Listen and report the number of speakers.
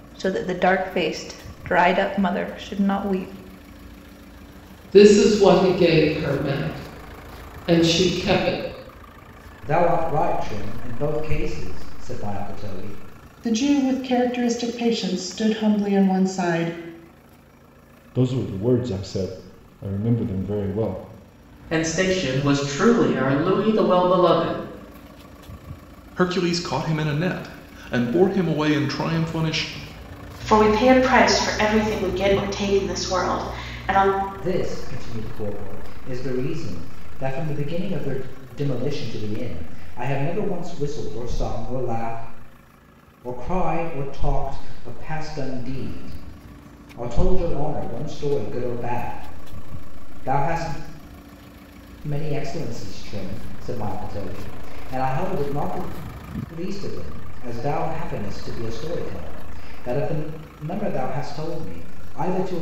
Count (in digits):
8